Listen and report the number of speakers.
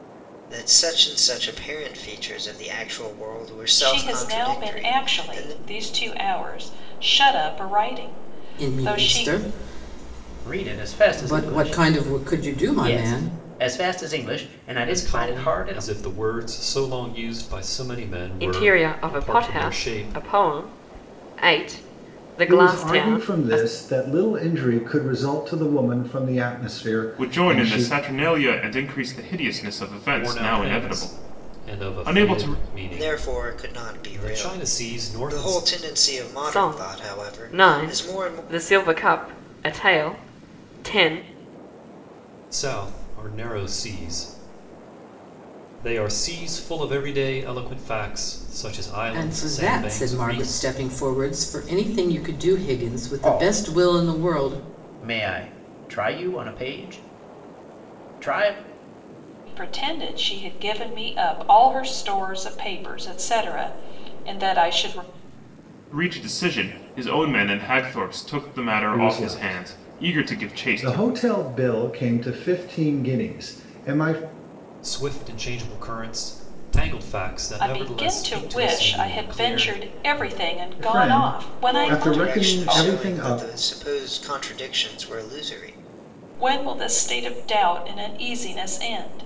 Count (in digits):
8